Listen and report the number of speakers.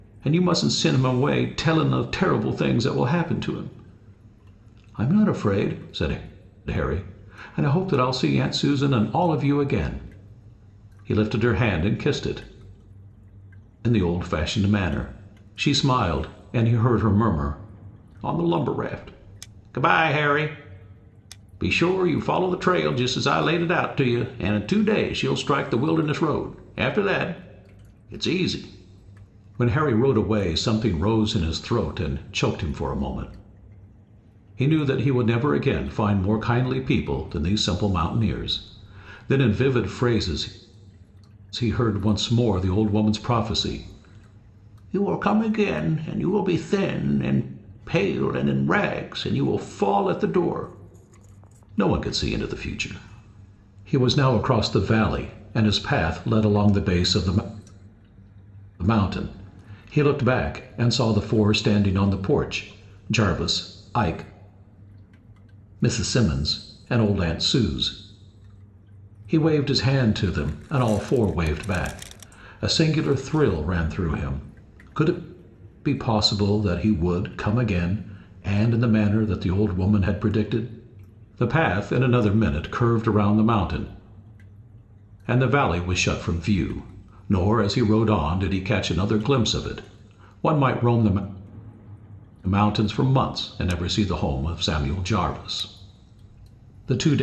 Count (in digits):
1